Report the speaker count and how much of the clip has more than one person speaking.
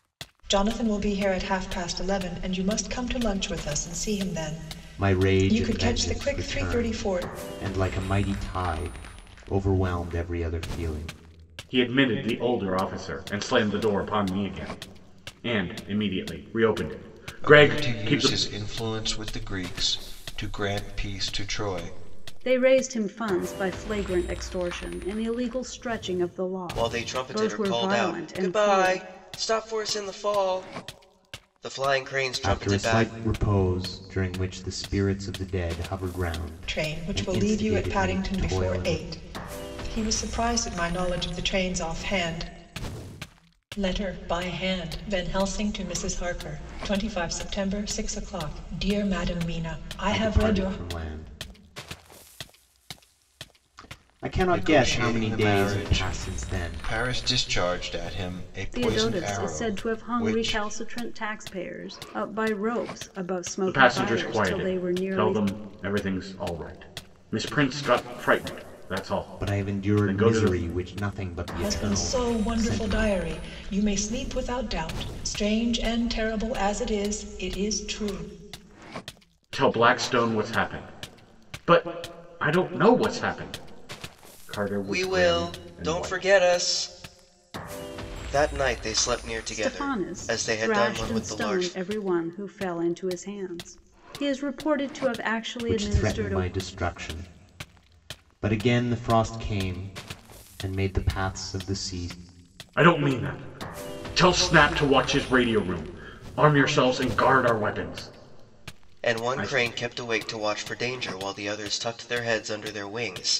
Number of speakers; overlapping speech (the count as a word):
six, about 21%